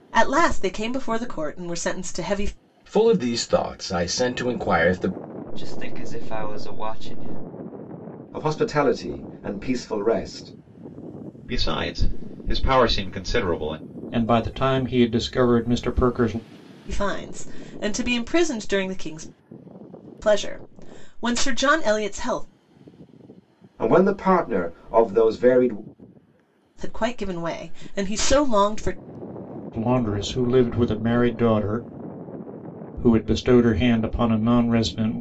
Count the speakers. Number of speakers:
six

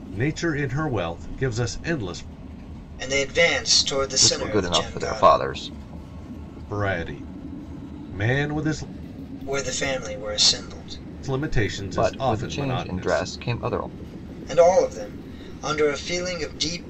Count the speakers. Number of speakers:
three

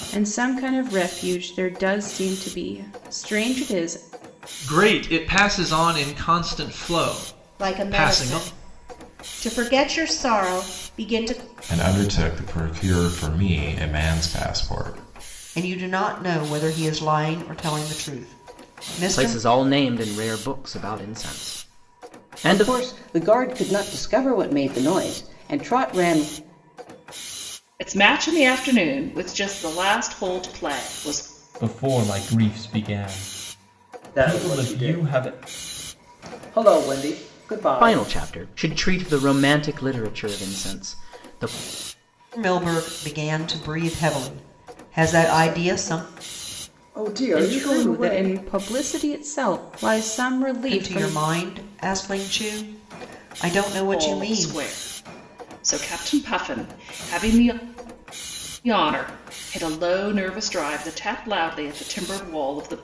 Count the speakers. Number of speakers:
ten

